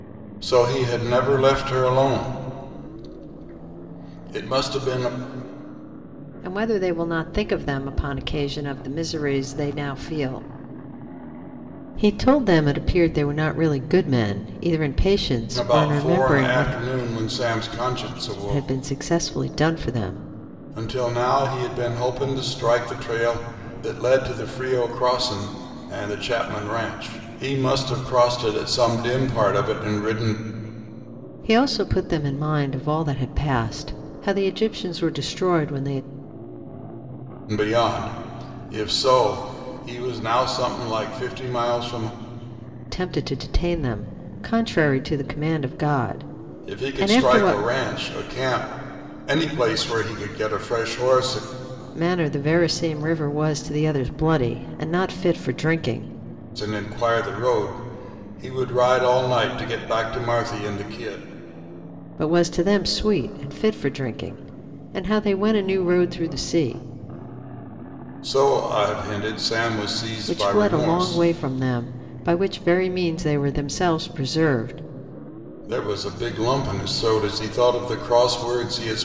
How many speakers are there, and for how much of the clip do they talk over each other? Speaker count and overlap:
two, about 5%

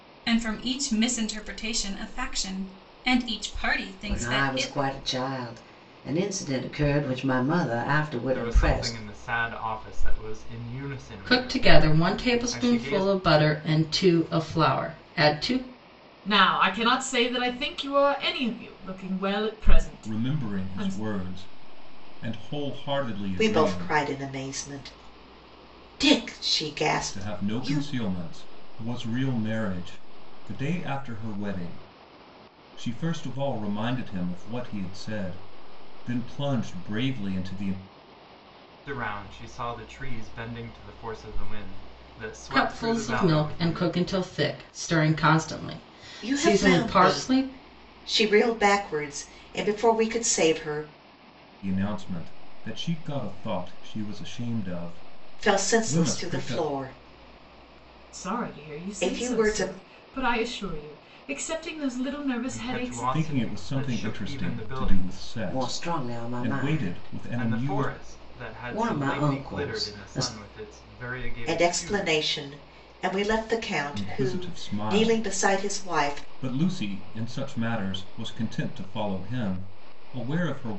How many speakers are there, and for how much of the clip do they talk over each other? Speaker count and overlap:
seven, about 28%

